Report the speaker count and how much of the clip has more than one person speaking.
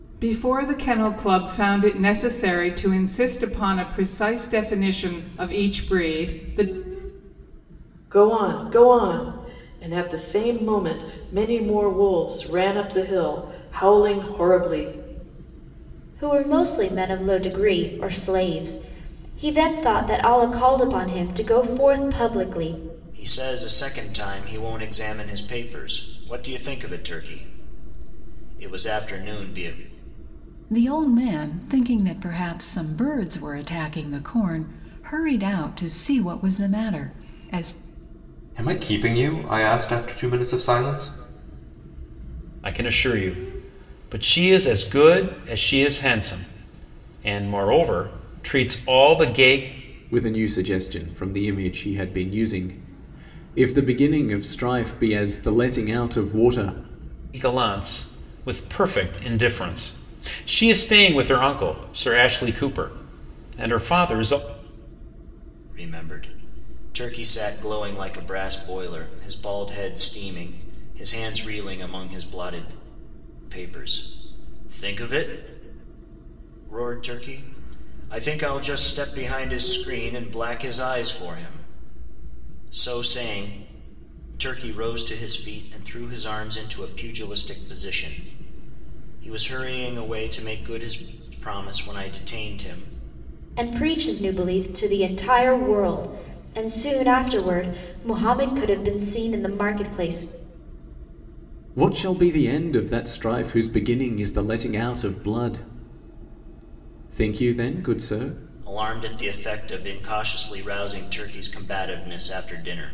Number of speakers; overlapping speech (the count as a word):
eight, no overlap